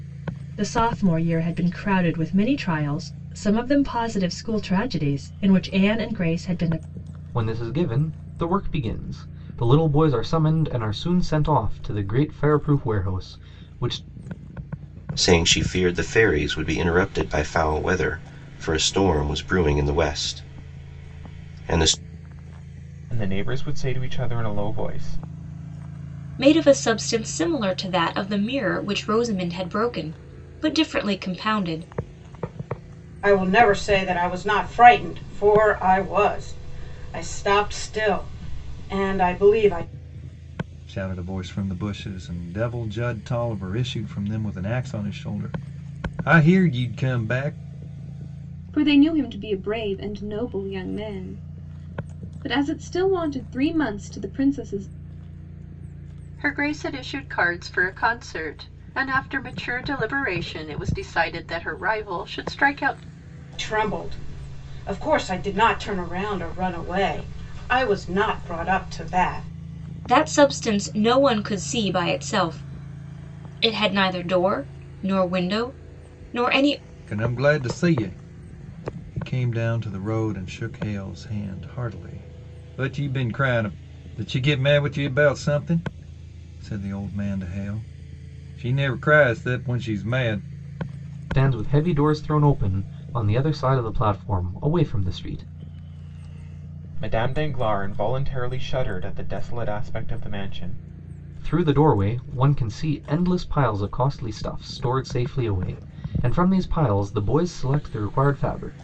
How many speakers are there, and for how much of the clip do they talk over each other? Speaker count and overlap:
nine, no overlap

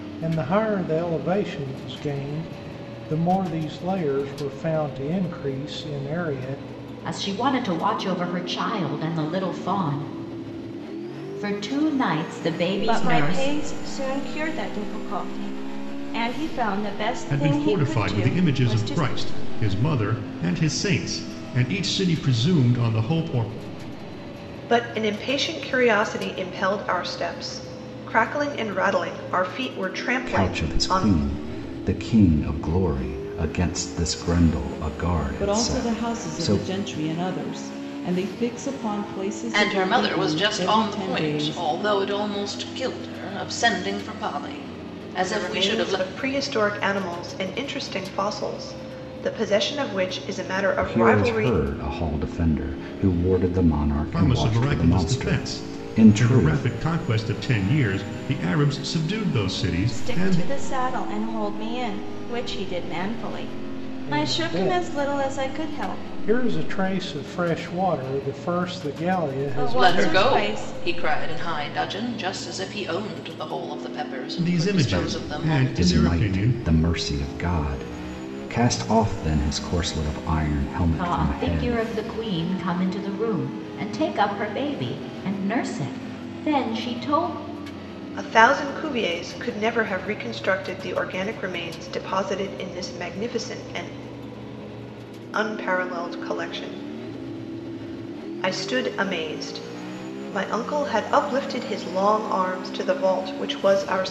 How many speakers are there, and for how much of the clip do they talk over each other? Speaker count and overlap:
eight, about 17%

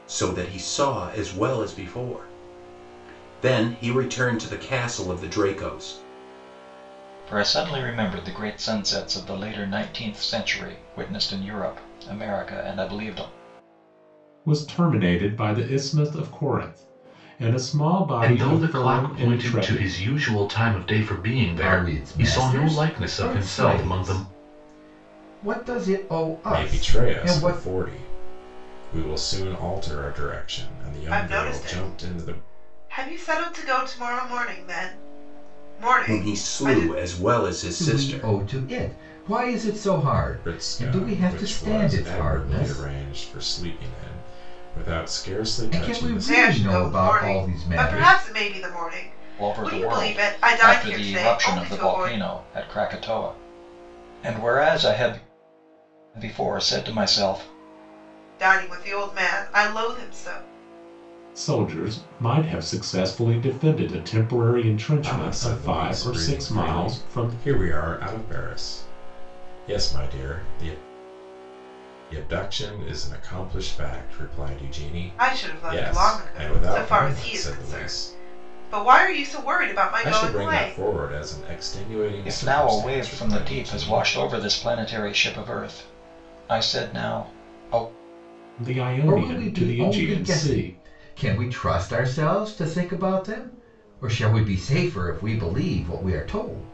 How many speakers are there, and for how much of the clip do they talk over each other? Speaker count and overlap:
seven, about 27%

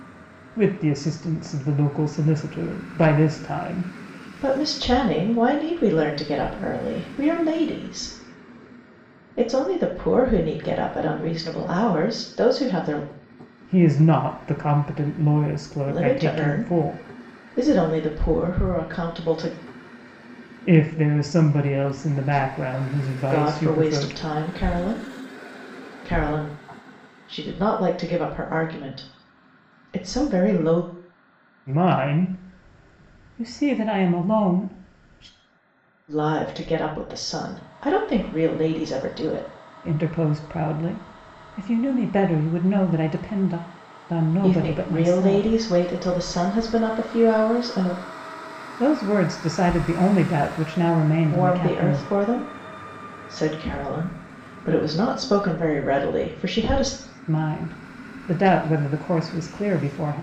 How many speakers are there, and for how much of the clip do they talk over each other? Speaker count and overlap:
two, about 7%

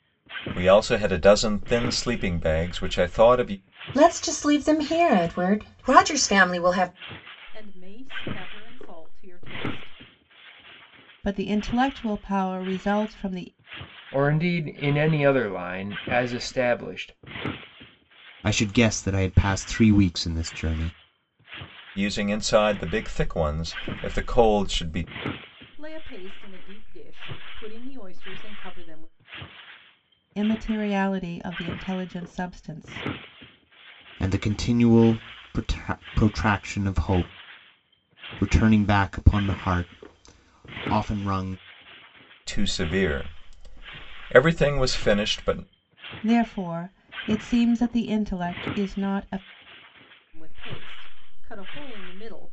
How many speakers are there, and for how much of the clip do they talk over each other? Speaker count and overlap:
six, no overlap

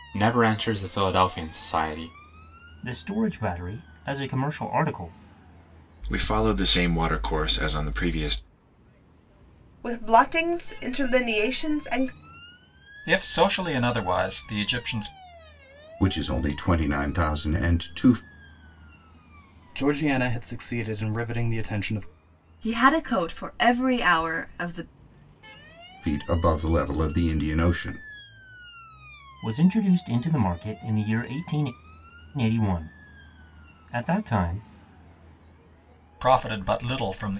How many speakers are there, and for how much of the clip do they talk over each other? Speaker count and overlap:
eight, no overlap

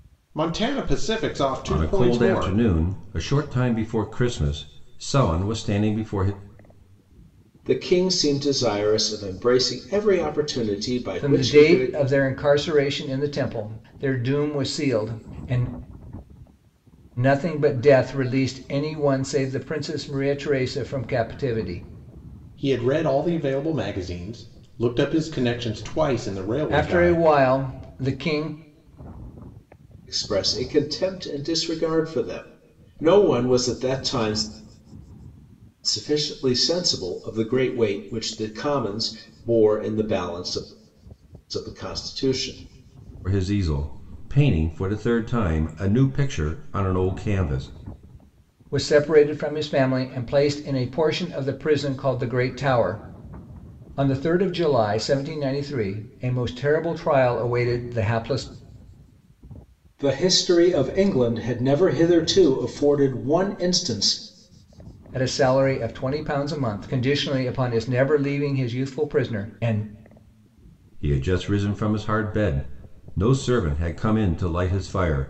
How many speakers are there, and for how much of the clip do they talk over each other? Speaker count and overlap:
four, about 3%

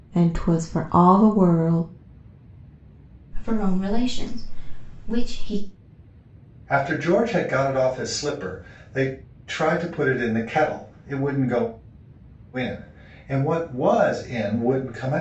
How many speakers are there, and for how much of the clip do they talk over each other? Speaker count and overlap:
three, no overlap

